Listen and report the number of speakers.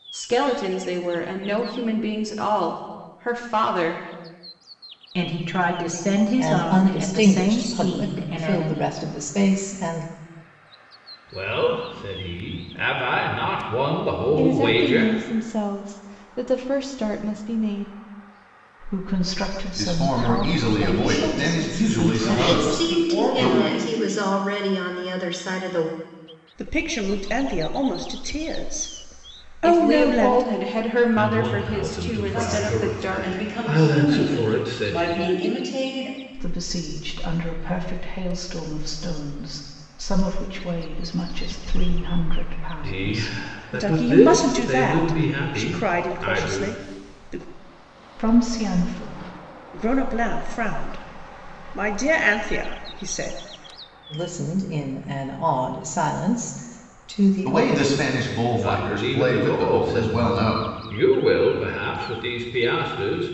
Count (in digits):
10